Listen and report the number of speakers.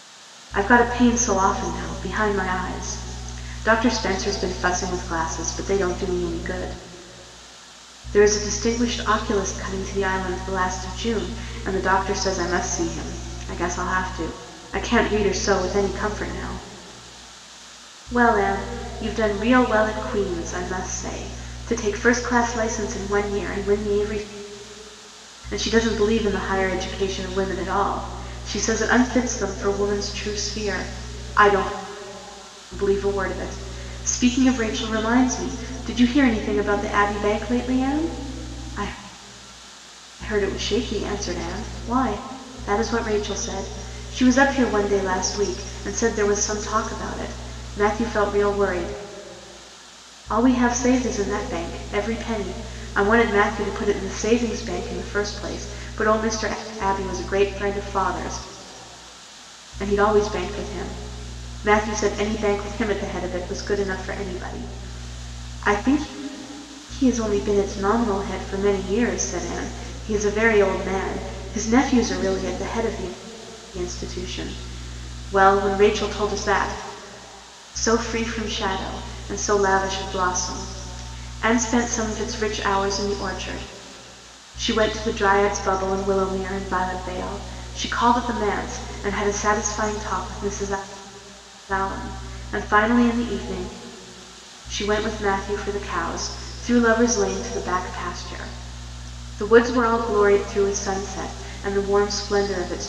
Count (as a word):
one